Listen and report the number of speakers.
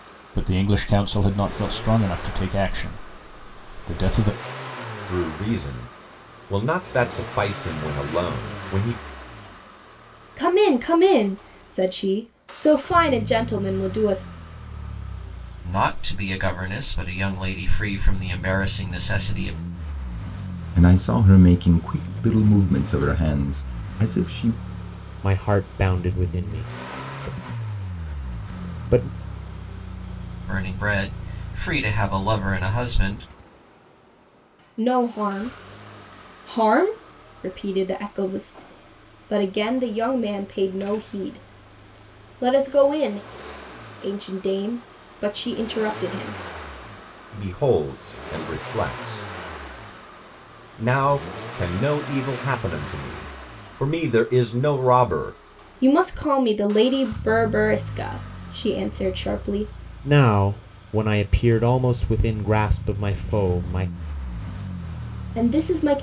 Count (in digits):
6